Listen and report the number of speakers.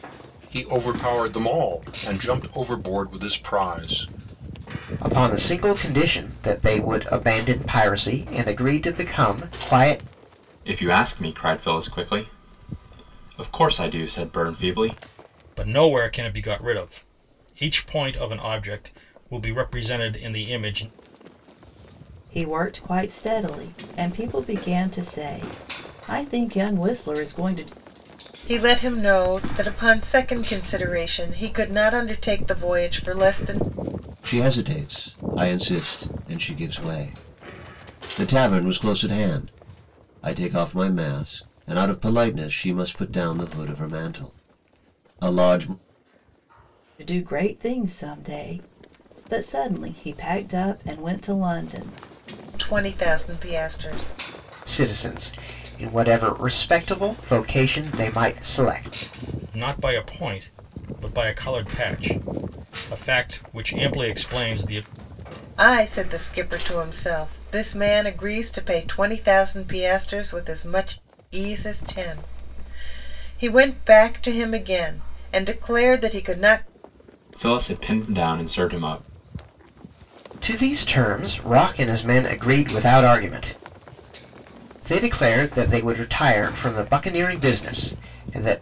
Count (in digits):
7